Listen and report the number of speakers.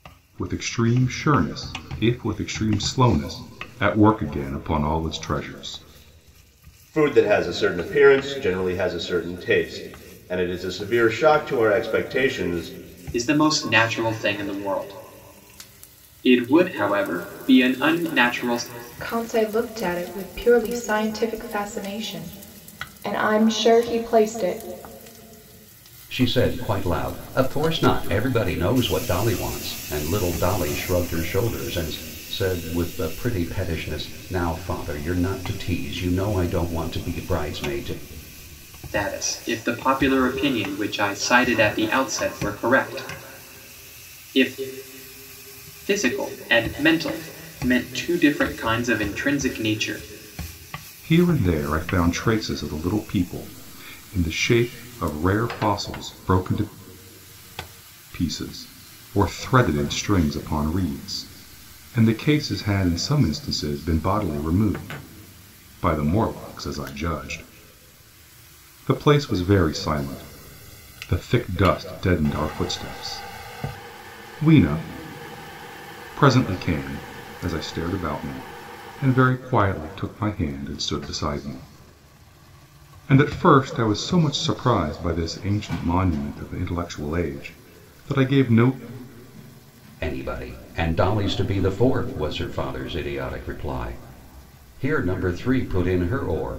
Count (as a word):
five